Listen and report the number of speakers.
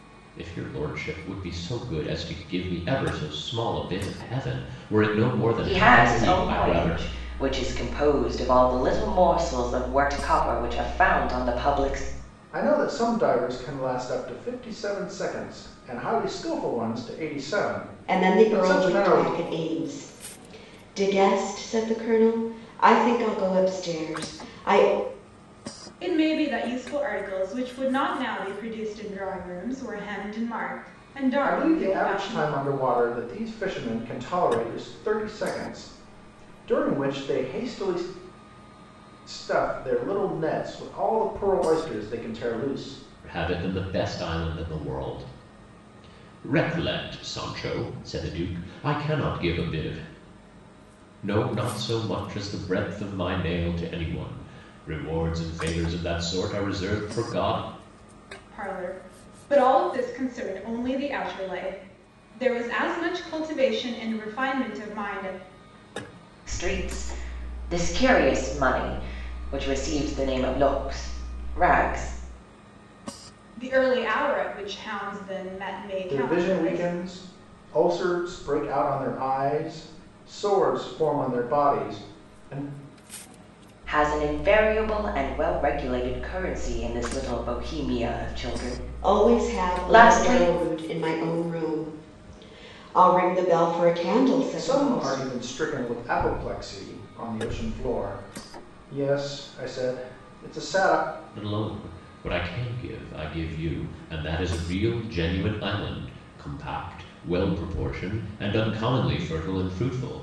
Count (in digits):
5